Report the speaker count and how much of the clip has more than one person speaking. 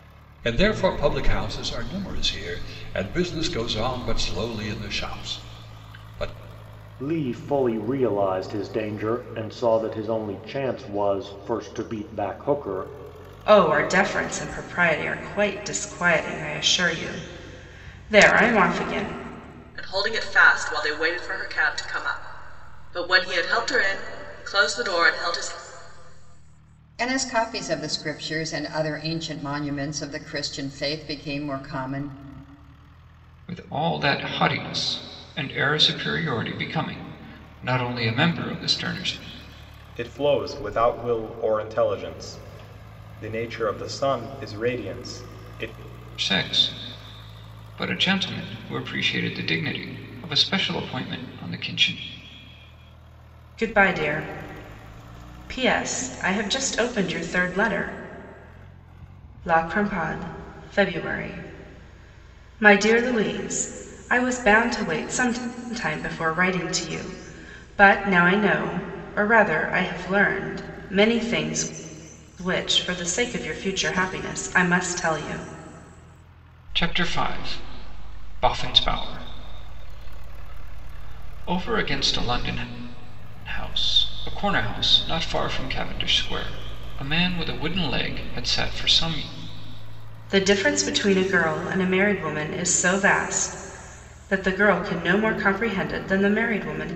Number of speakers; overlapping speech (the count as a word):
seven, no overlap